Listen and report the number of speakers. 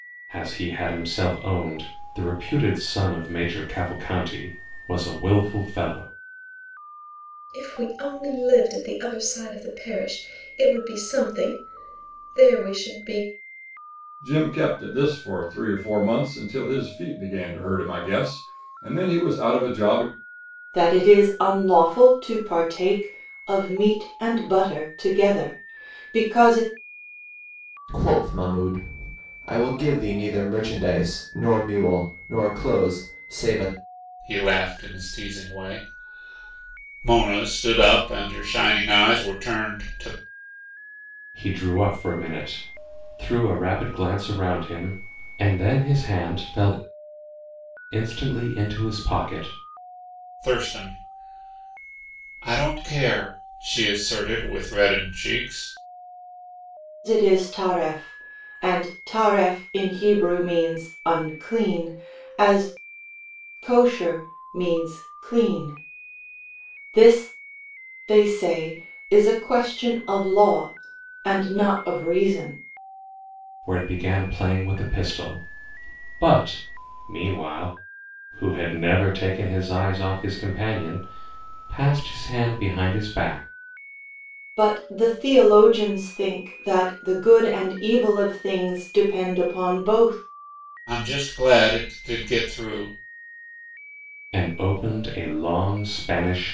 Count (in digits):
6